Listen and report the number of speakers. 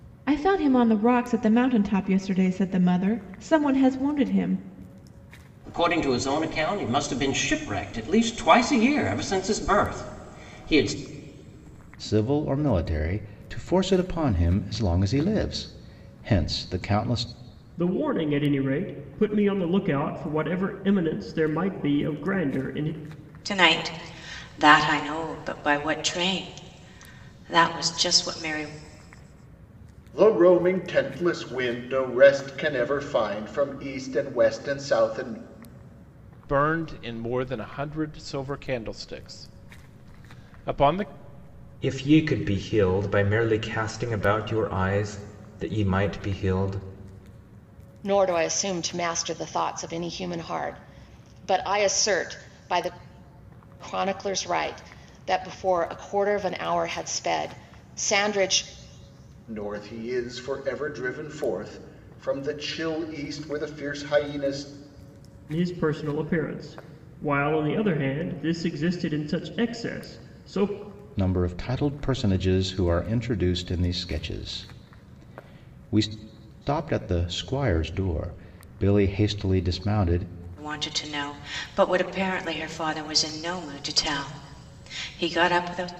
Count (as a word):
nine